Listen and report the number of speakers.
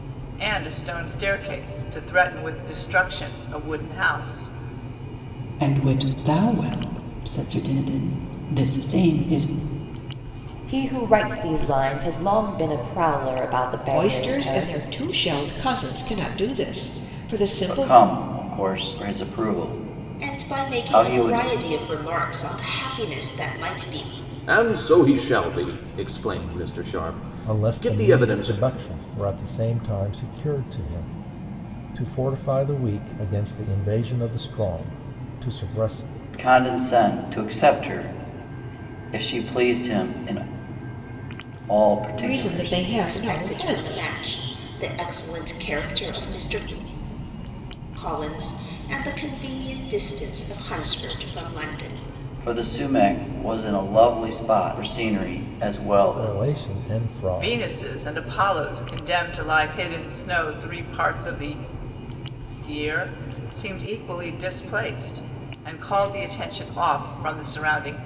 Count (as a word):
eight